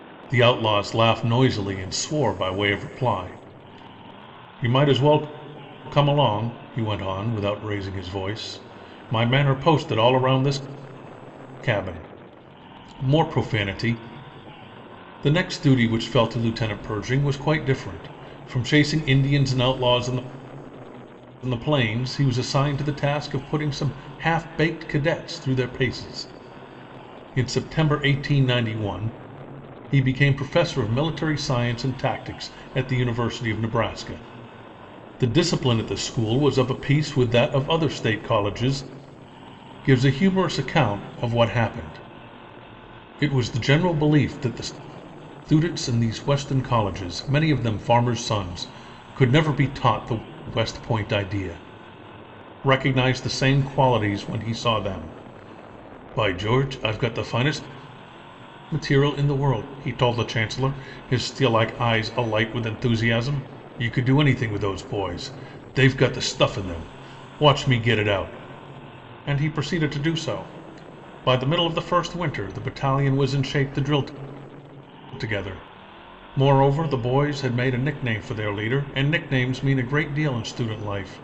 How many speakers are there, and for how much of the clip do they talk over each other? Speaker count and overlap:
one, no overlap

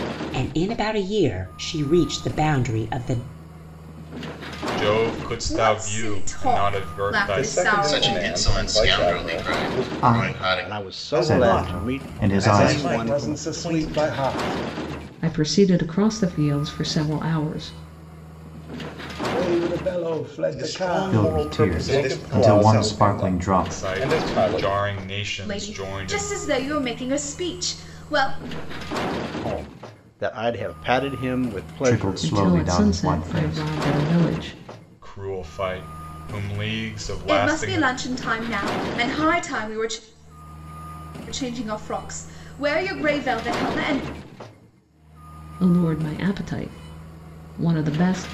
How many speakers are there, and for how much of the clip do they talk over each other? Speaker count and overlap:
ten, about 34%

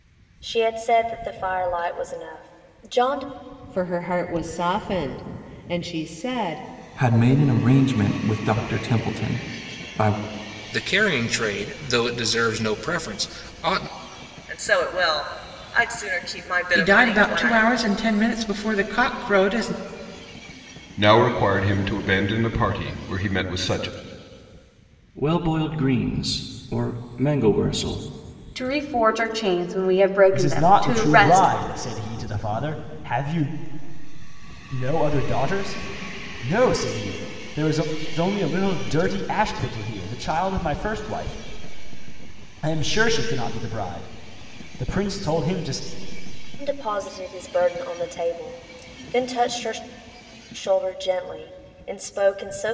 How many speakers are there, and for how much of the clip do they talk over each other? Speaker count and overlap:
ten, about 4%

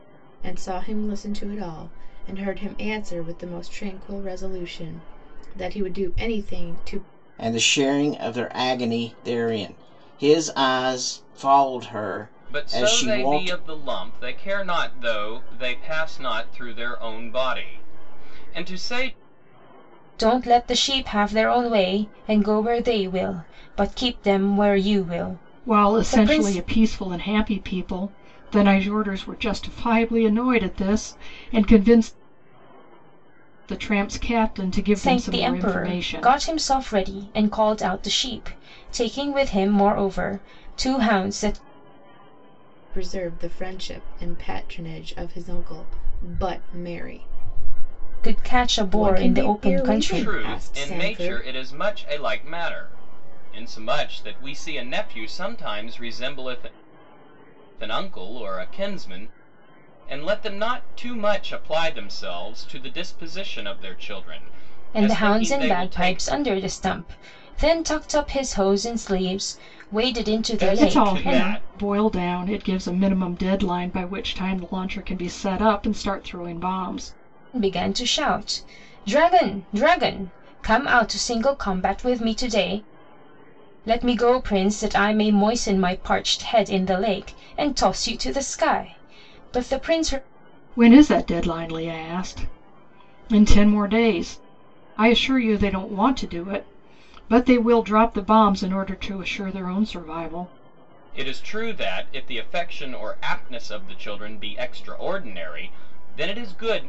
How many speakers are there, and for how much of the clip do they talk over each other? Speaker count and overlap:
five, about 9%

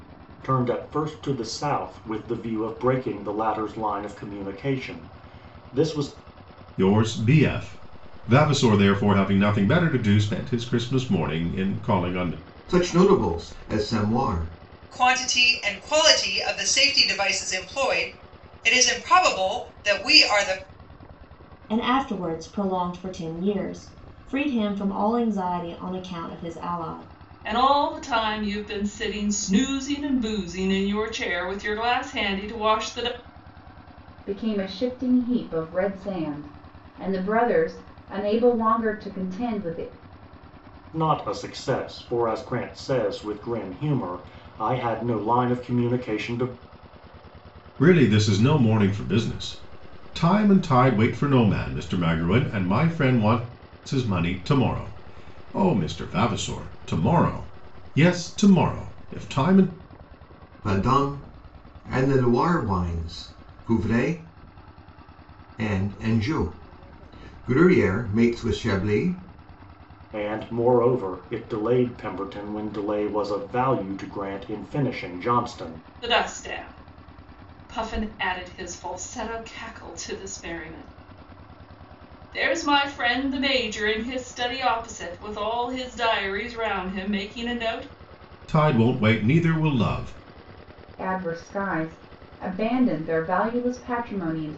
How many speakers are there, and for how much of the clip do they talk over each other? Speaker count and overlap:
seven, no overlap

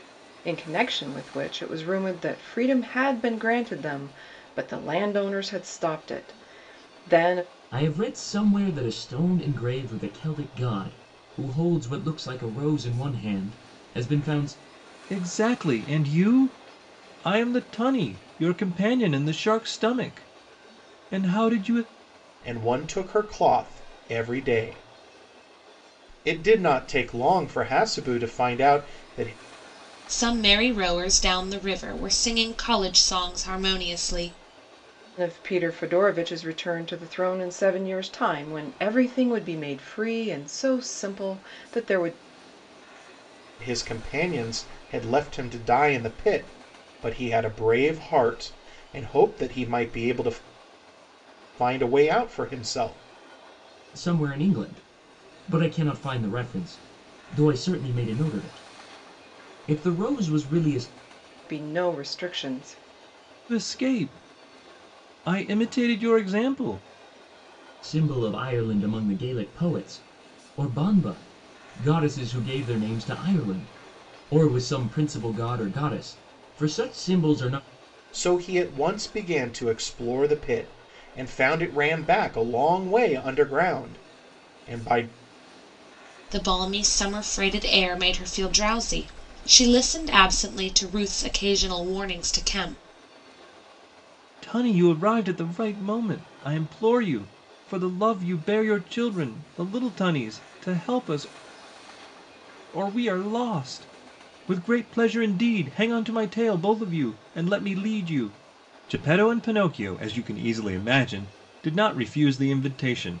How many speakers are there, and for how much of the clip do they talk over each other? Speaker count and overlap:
five, no overlap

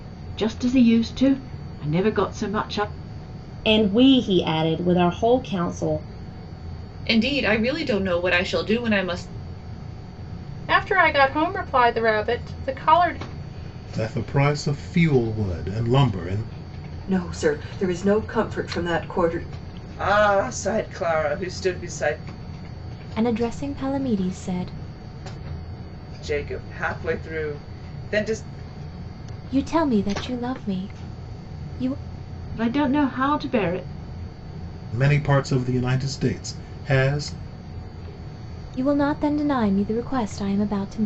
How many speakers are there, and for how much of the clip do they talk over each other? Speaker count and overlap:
eight, no overlap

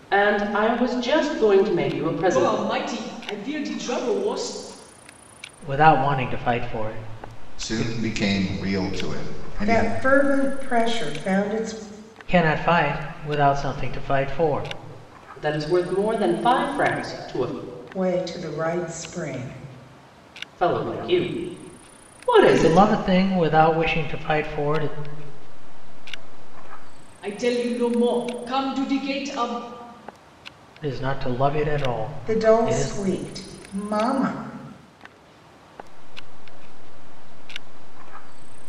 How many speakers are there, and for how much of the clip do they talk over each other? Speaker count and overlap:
six, about 12%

